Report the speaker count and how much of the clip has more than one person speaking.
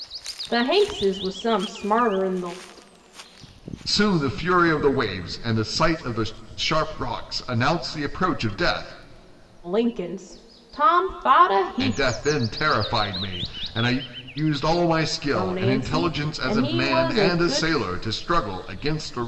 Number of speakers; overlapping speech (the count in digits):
2, about 14%